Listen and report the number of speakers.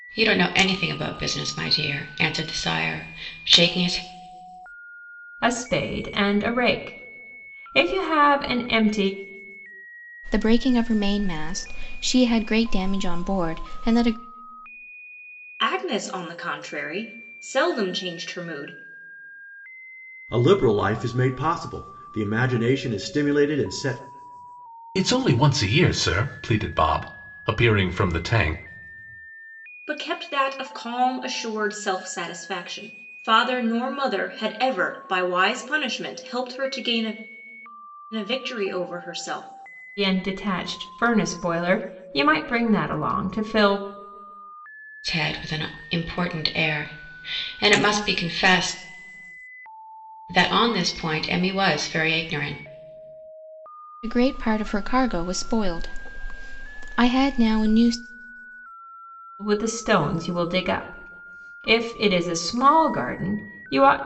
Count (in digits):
6